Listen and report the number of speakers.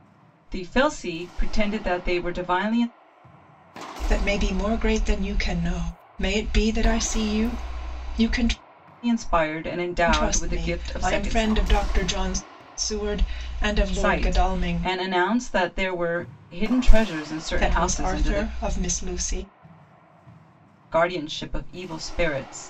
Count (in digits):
2